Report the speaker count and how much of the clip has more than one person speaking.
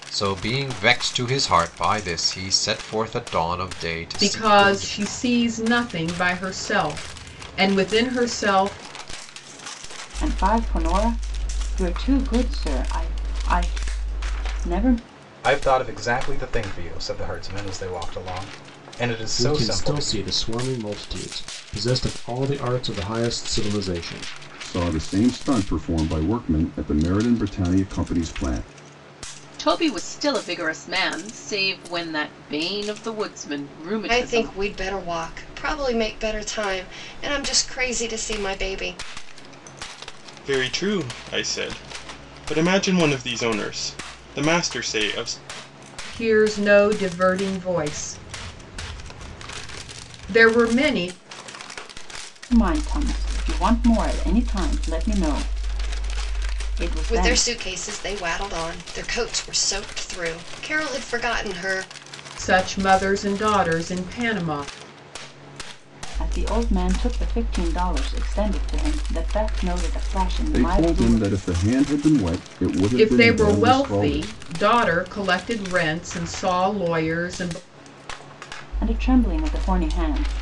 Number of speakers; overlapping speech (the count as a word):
nine, about 6%